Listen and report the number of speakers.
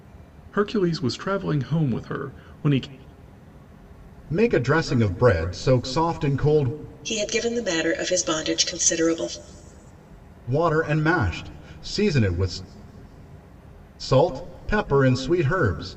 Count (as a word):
three